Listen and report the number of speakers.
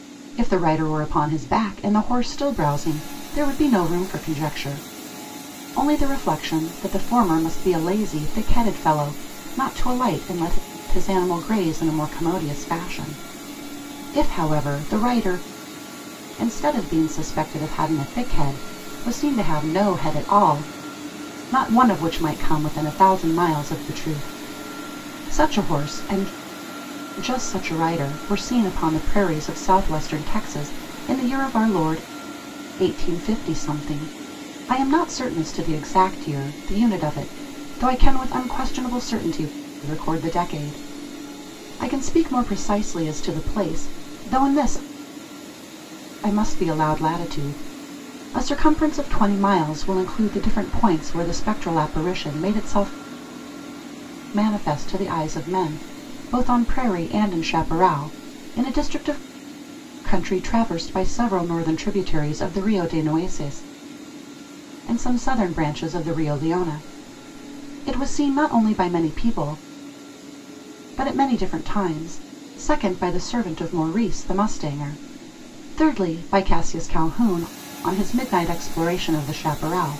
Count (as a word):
one